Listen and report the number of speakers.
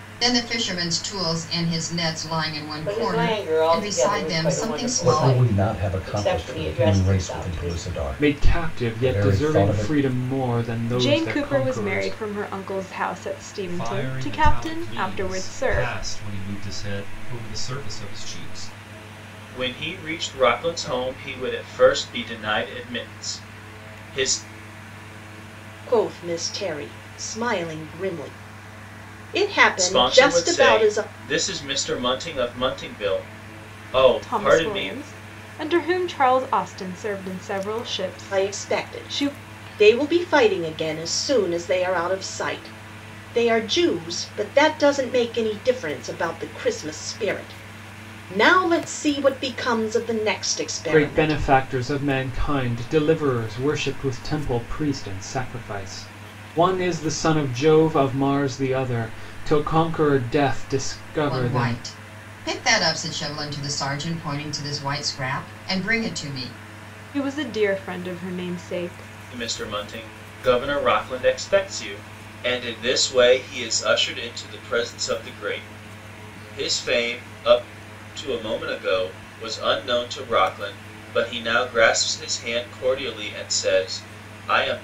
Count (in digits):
8